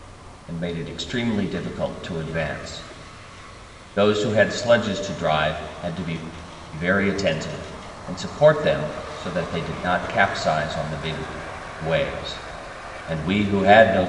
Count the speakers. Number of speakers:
1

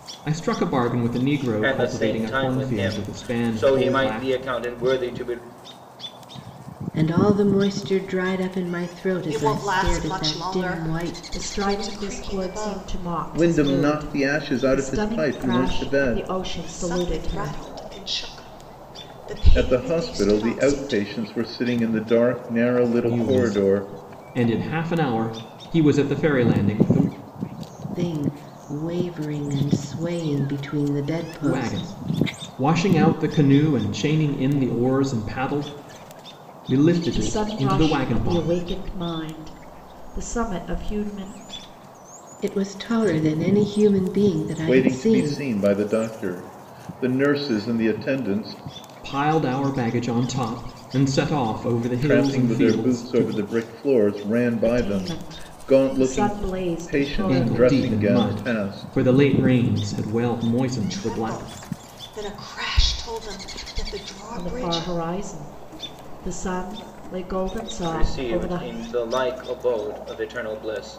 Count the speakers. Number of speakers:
6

